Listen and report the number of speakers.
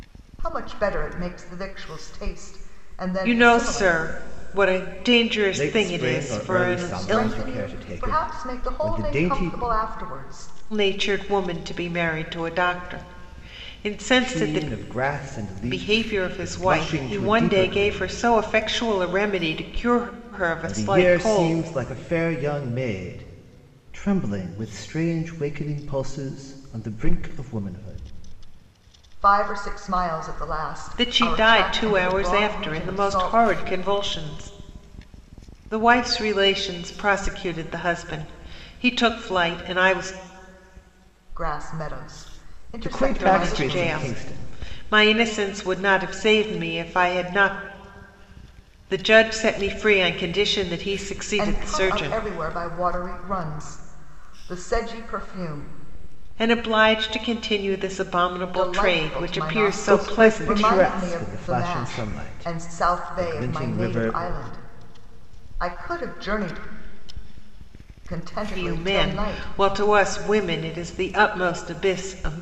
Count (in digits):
3